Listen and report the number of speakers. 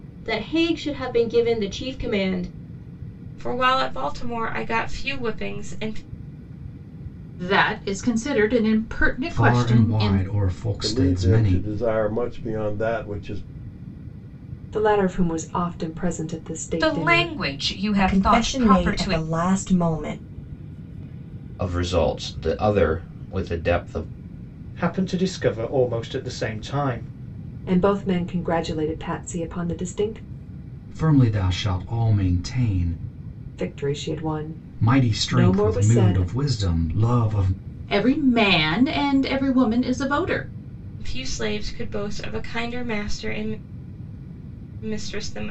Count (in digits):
10